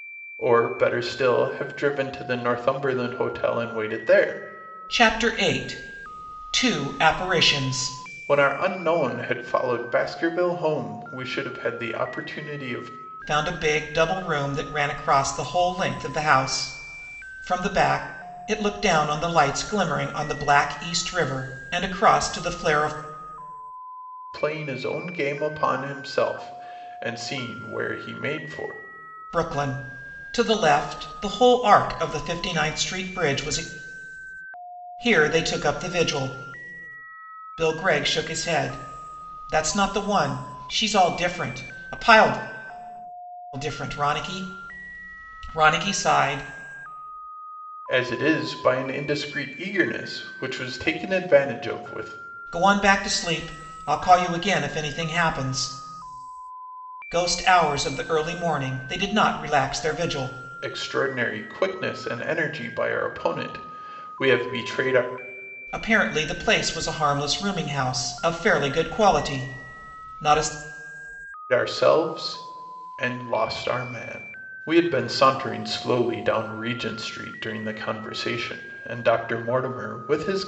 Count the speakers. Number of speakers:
2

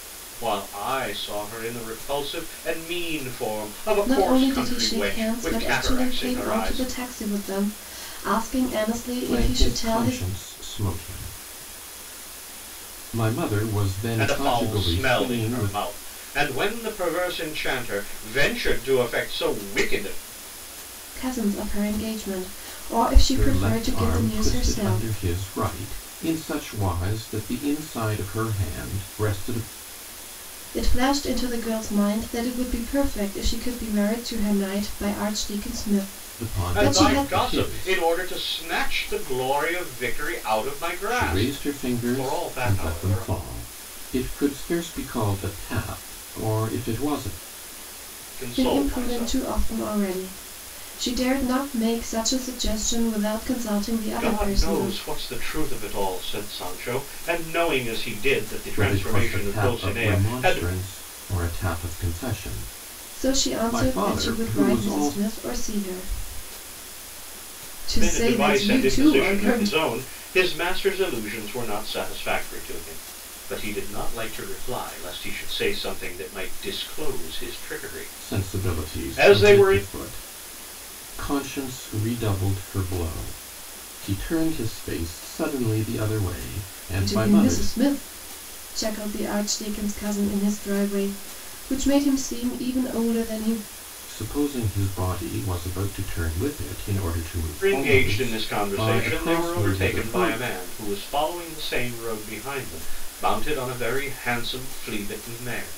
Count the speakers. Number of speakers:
3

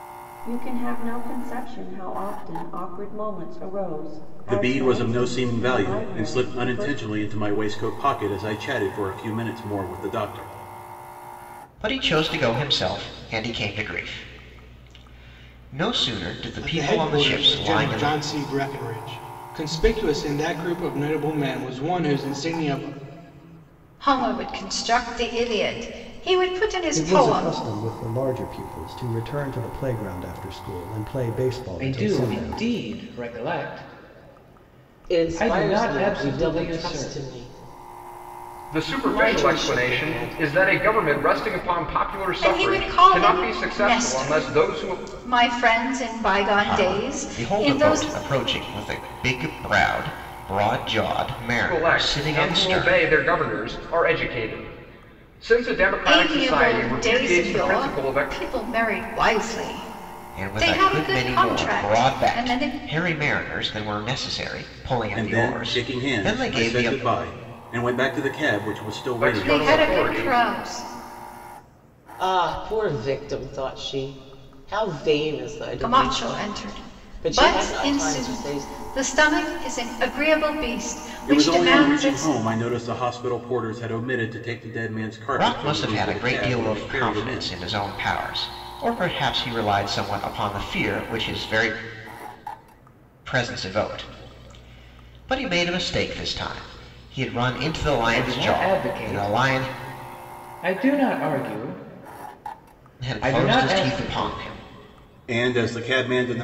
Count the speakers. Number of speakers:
9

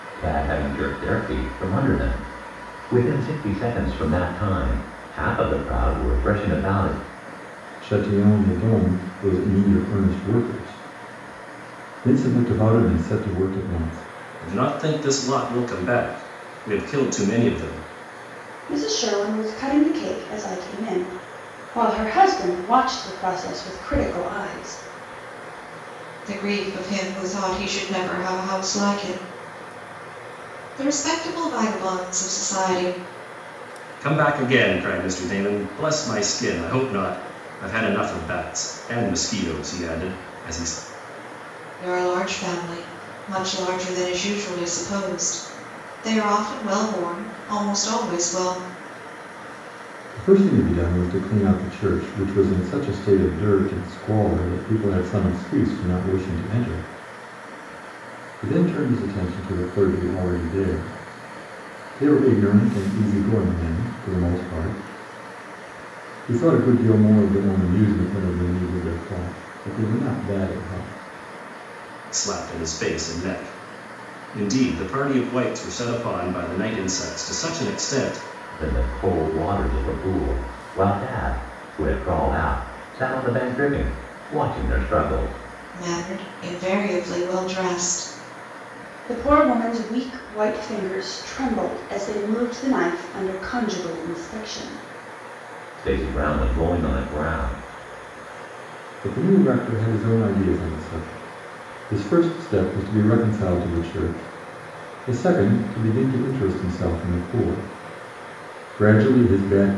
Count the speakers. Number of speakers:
5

